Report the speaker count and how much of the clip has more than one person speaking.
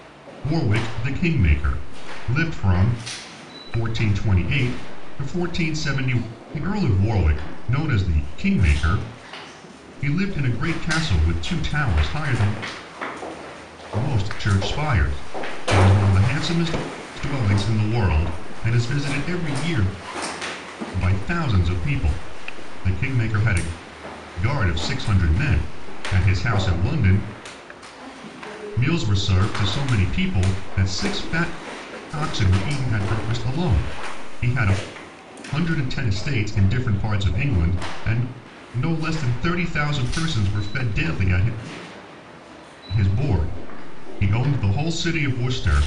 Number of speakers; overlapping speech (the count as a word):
one, no overlap